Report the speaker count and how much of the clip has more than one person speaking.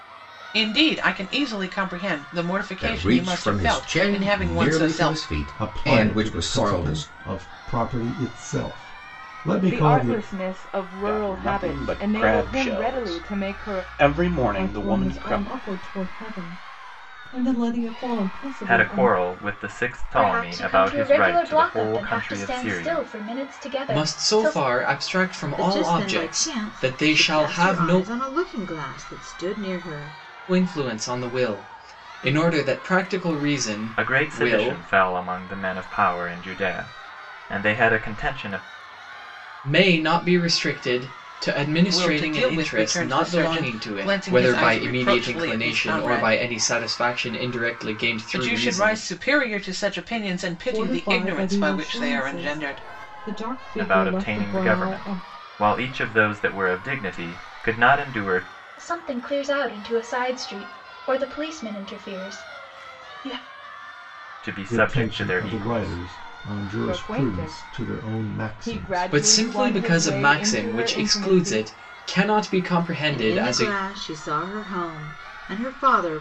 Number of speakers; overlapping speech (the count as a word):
ten, about 42%